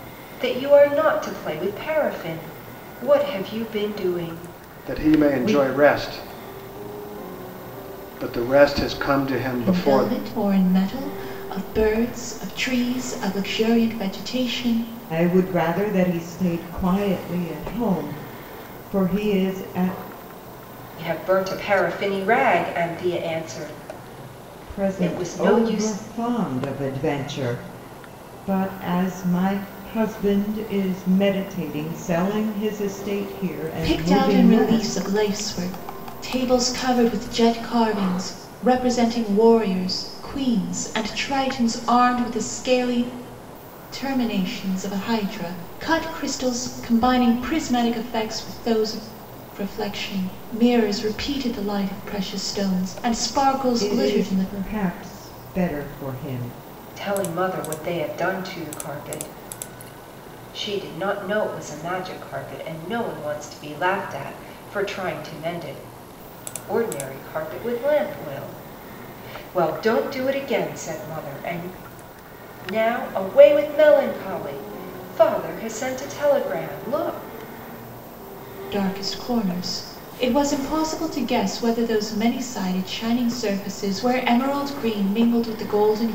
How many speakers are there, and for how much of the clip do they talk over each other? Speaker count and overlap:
four, about 6%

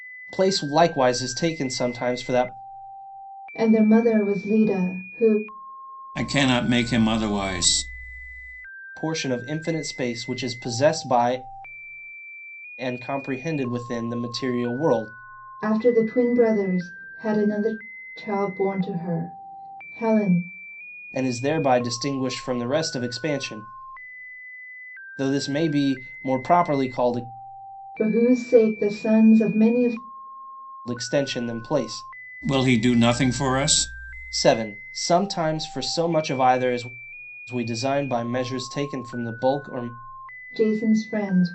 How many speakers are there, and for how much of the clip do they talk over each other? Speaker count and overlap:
three, no overlap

